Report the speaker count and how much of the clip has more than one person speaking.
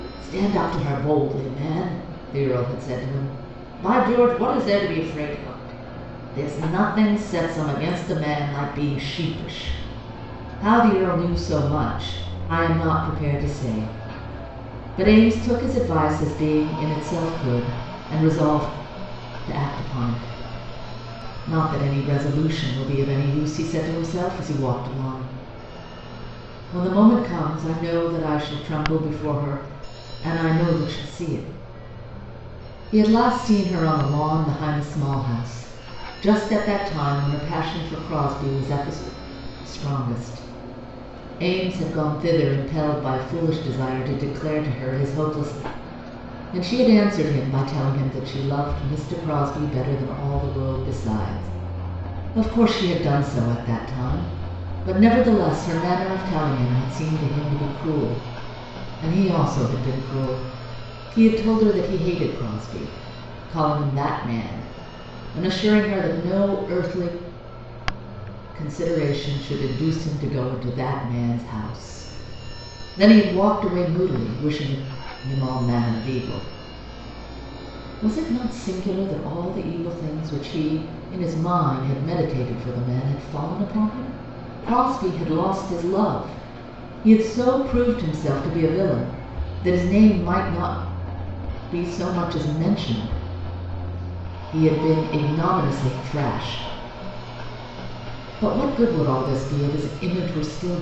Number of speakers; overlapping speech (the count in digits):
1, no overlap